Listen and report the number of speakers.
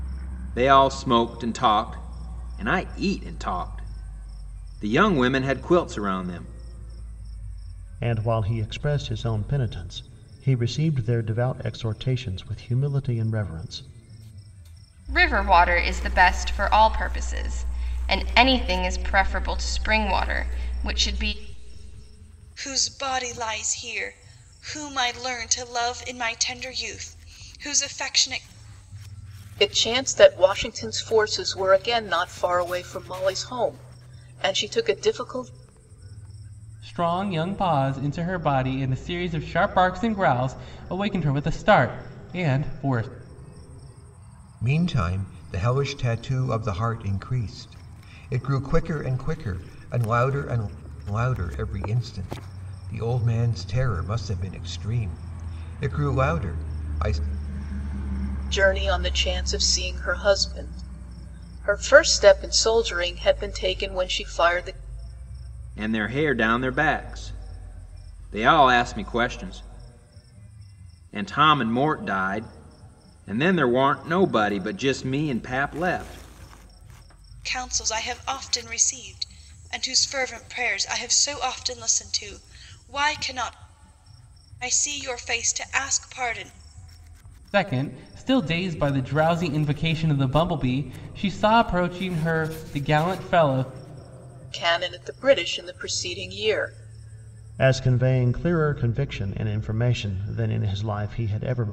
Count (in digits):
7